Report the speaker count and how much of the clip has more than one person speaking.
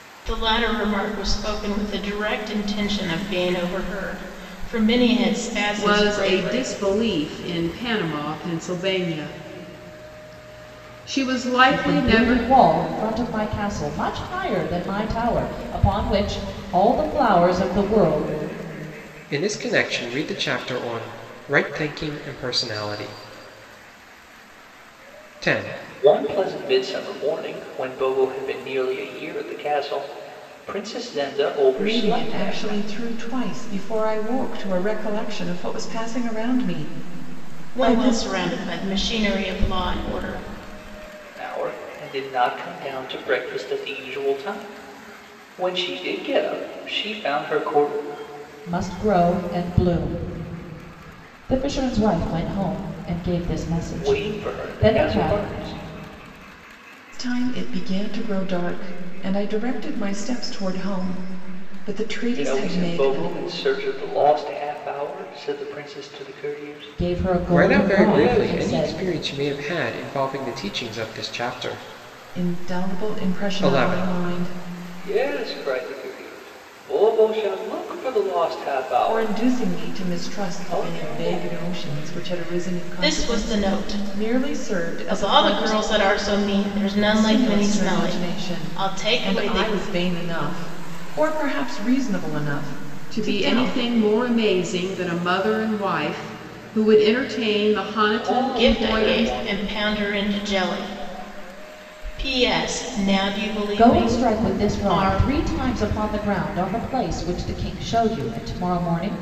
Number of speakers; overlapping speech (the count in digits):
6, about 19%